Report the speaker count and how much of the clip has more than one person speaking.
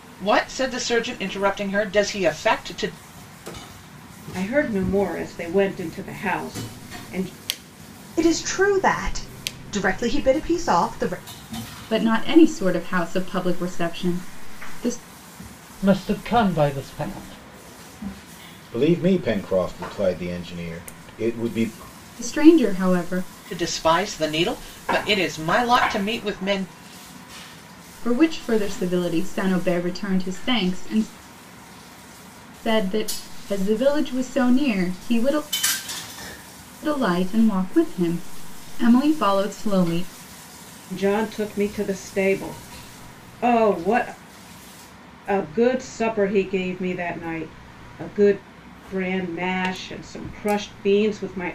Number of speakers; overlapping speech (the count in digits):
6, no overlap